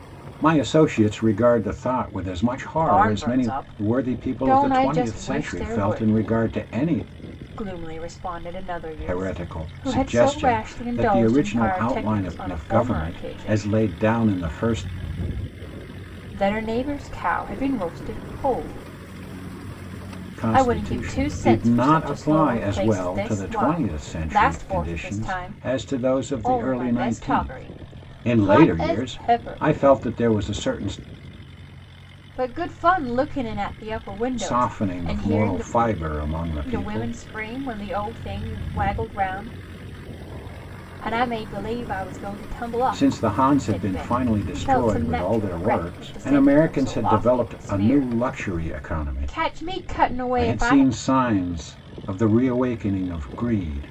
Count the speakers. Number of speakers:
two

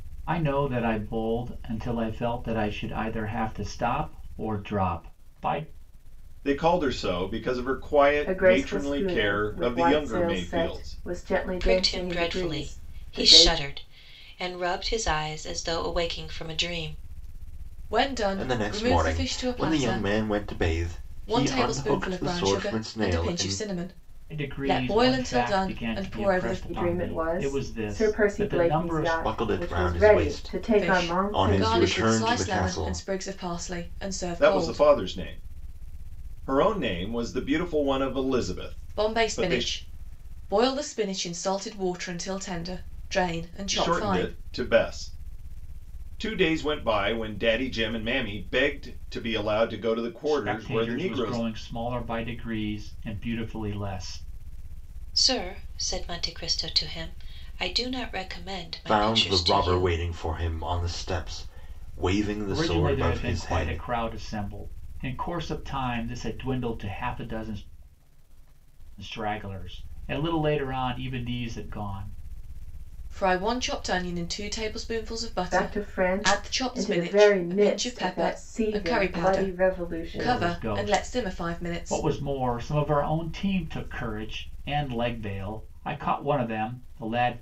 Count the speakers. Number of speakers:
six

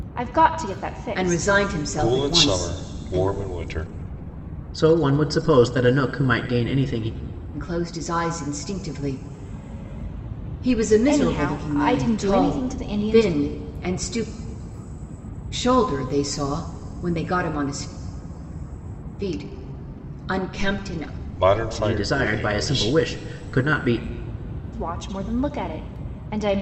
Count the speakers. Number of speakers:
four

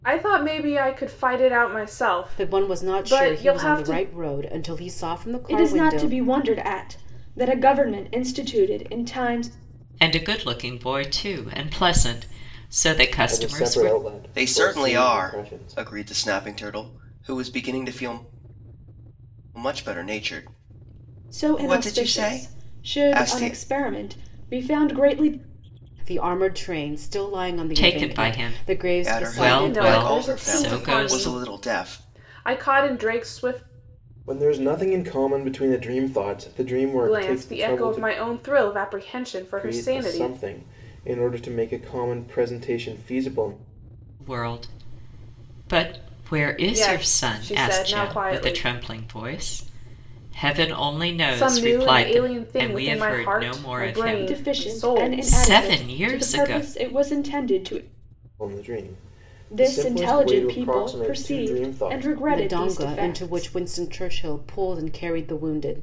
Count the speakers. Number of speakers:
six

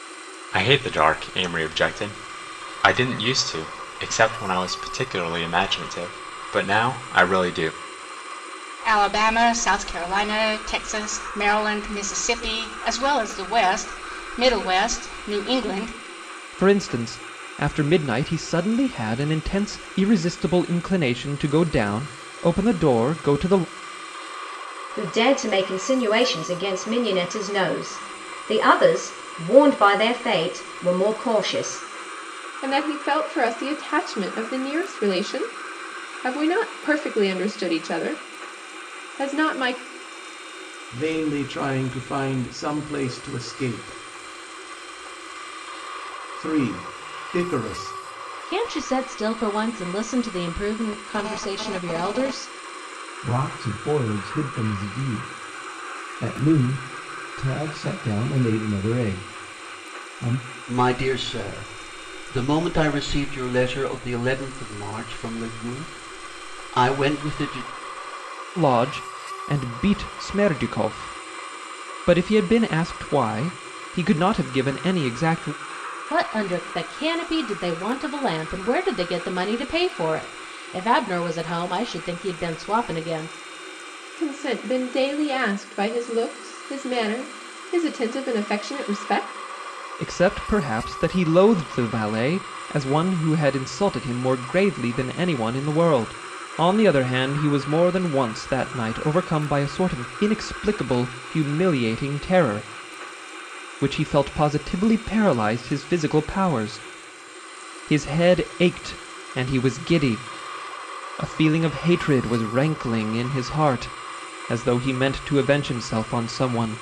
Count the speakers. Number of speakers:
nine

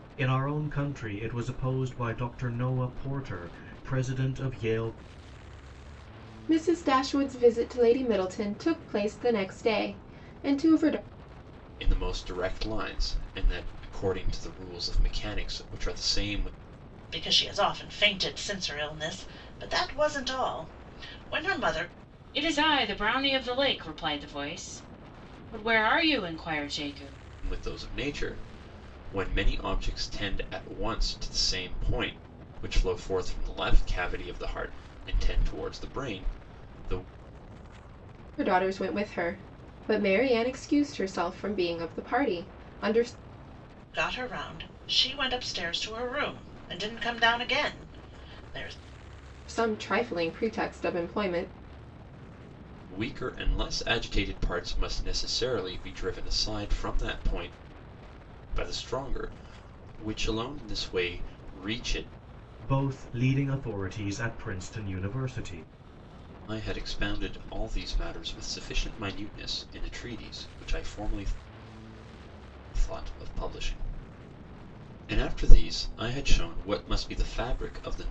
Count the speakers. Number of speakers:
five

